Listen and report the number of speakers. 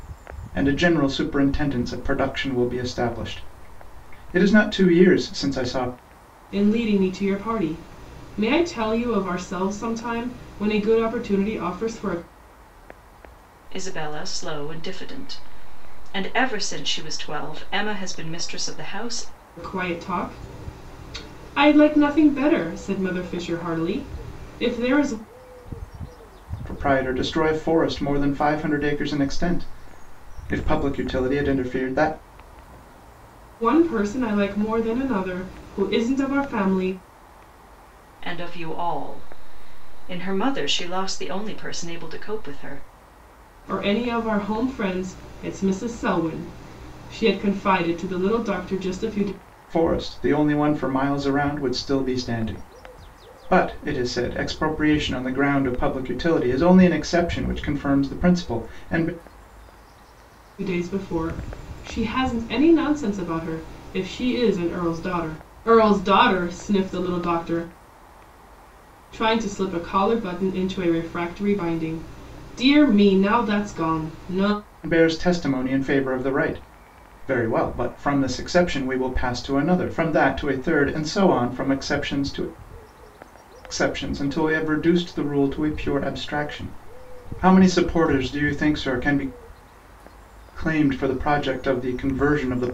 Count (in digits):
3